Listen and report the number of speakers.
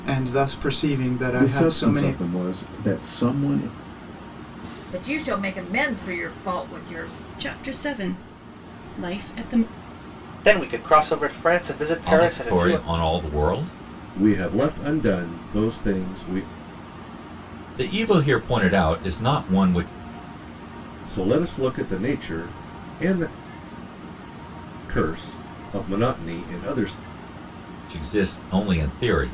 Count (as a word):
seven